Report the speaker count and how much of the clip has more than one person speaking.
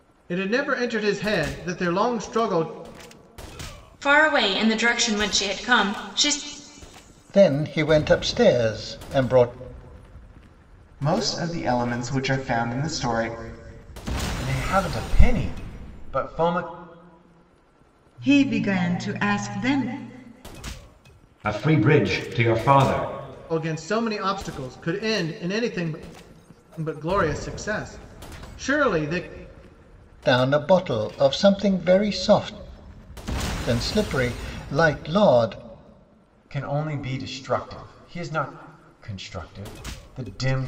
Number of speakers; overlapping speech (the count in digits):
7, no overlap